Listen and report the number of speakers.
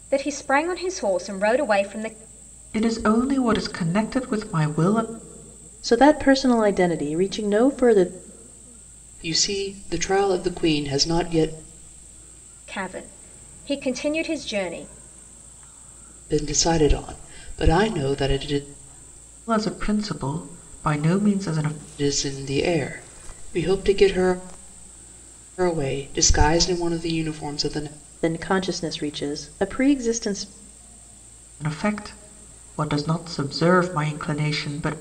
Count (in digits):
4